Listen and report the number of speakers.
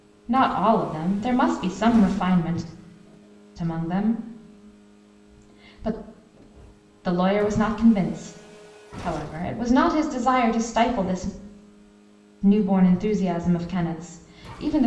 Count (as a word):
one